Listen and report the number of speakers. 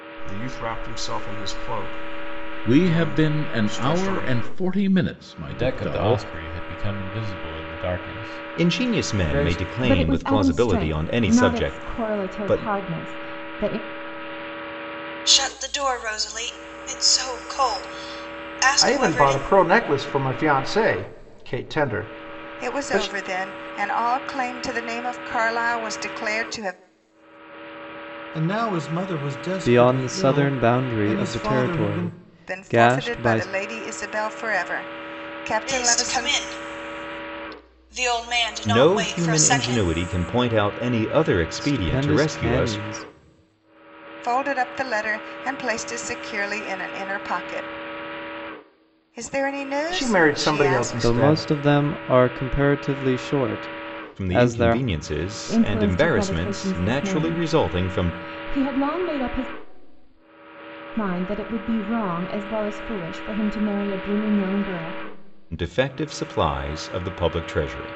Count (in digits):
10